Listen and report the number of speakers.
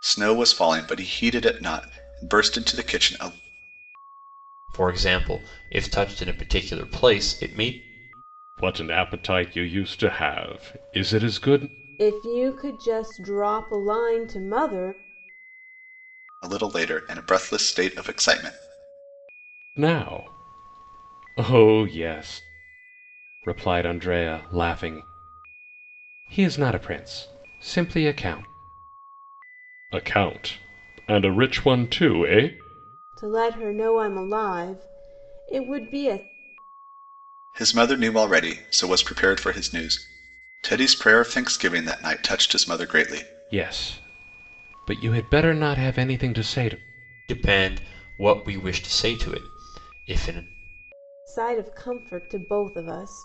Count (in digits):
4